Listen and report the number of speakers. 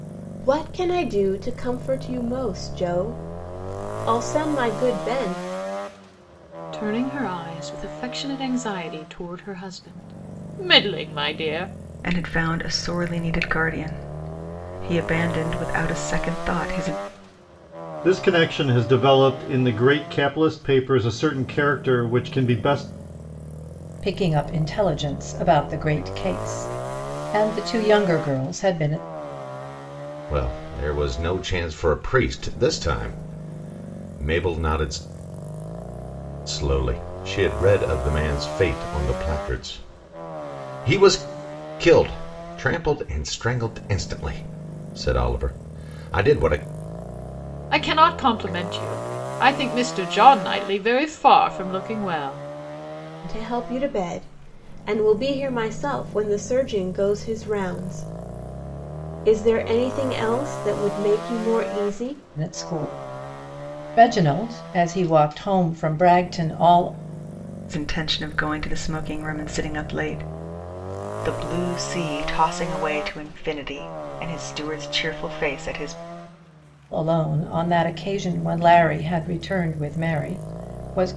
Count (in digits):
6